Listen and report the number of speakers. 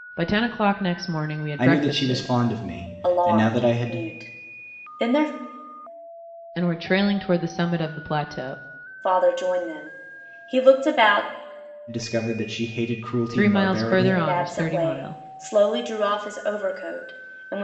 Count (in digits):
3